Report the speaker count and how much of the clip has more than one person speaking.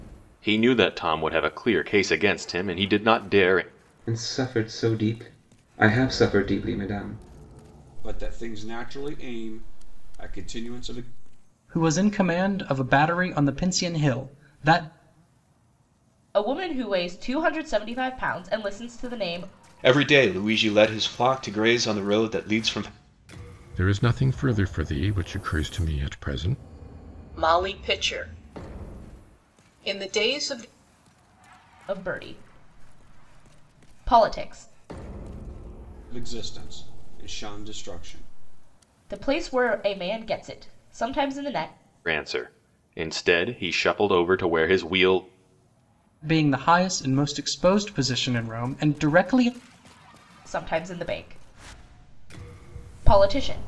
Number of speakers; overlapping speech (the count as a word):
eight, no overlap